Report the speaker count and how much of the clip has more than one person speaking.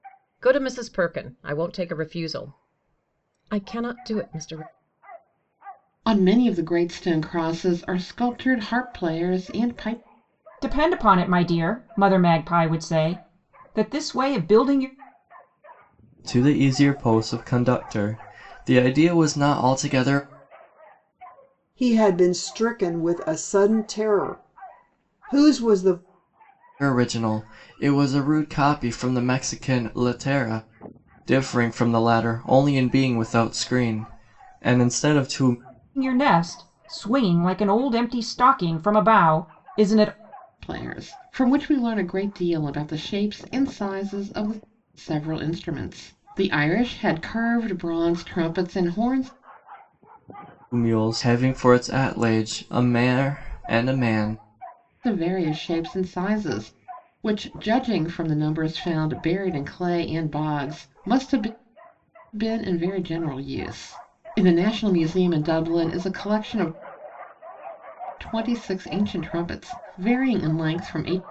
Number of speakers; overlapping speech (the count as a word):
five, no overlap